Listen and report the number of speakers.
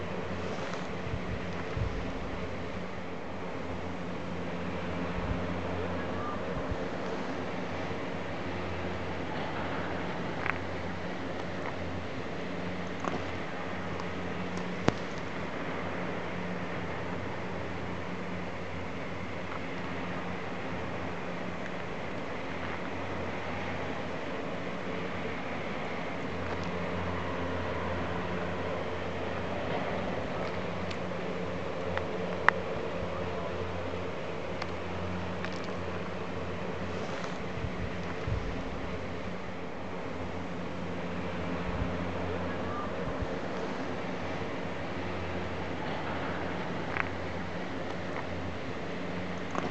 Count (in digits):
0